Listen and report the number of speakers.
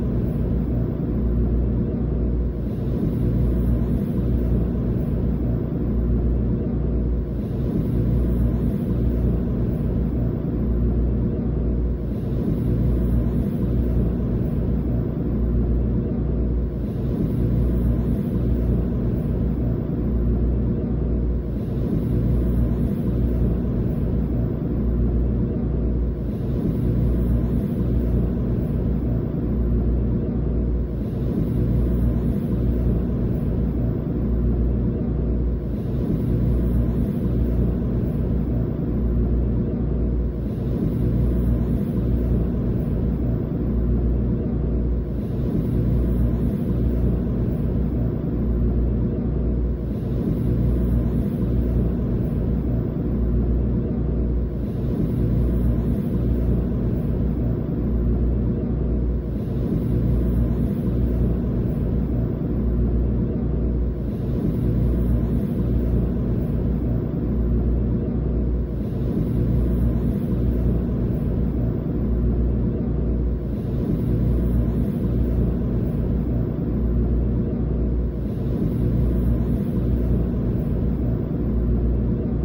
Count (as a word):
zero